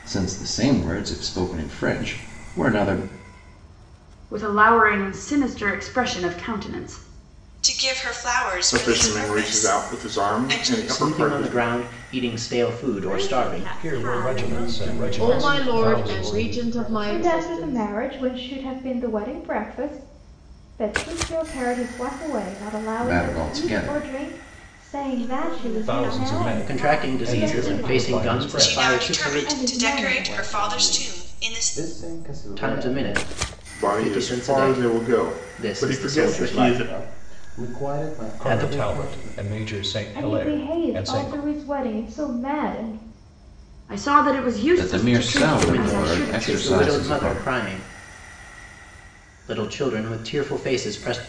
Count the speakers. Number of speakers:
10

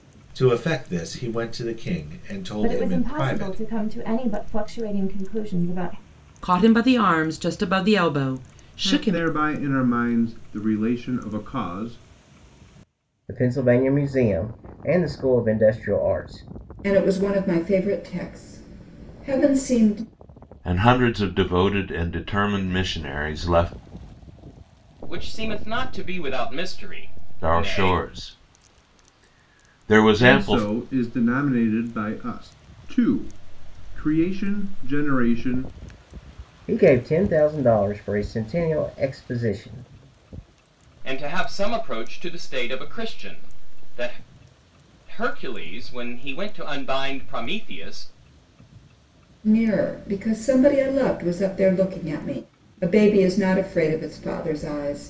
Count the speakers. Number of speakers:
8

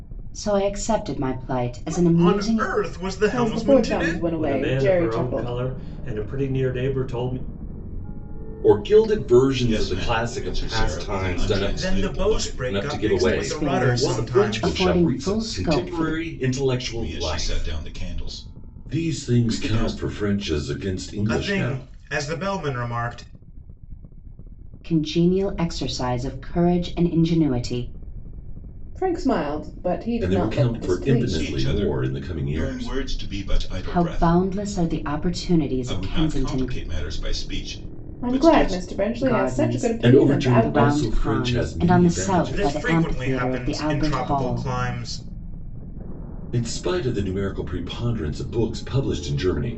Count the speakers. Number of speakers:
6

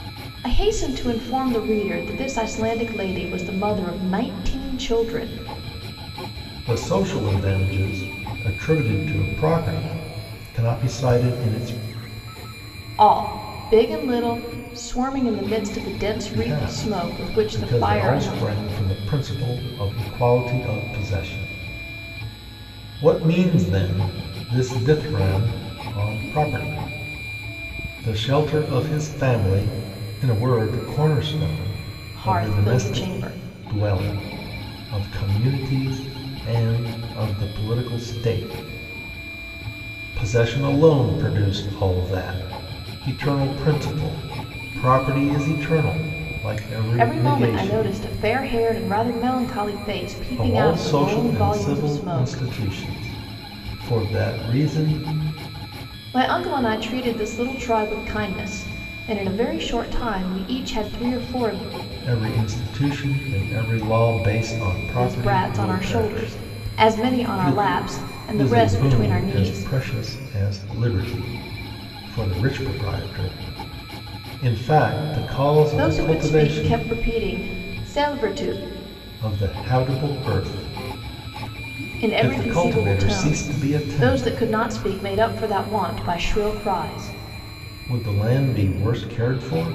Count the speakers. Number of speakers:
2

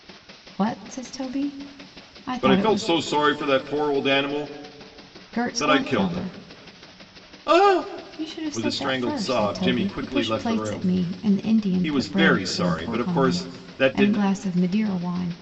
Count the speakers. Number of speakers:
2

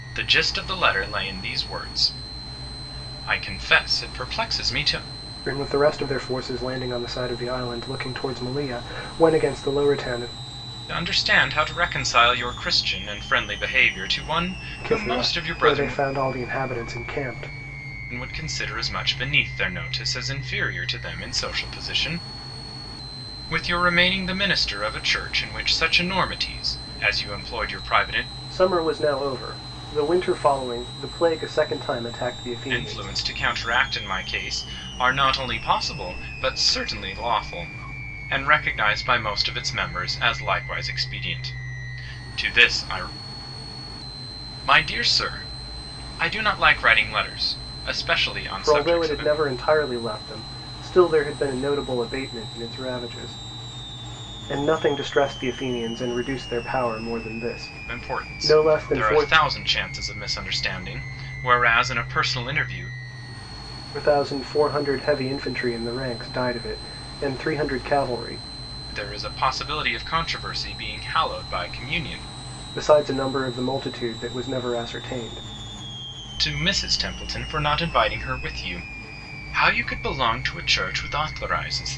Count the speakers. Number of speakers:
2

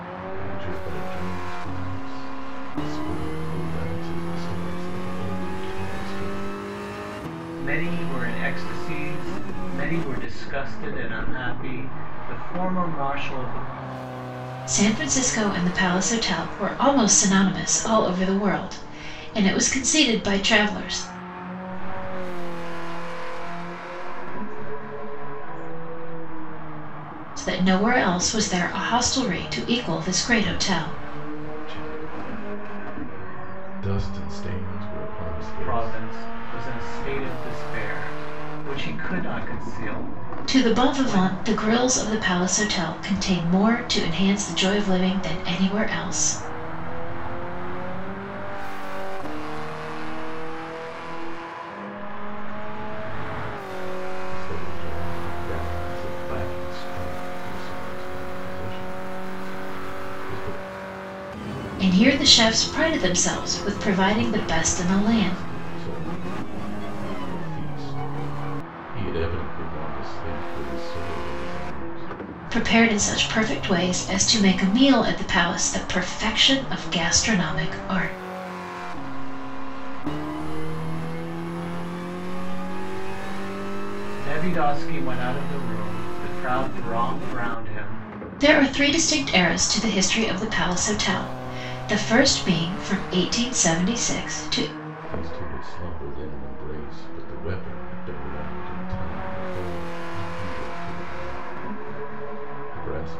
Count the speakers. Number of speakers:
4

